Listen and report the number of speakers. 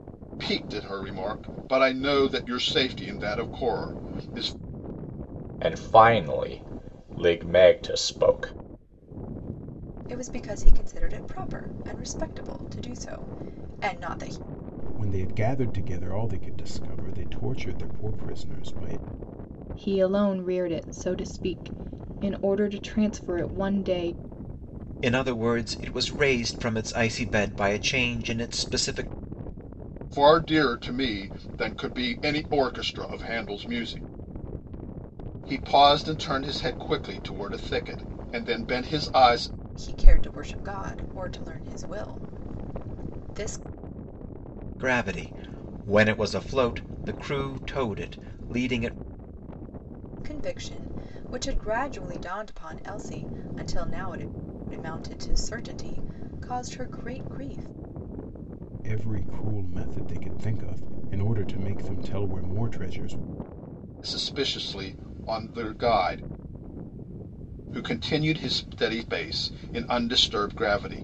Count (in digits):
6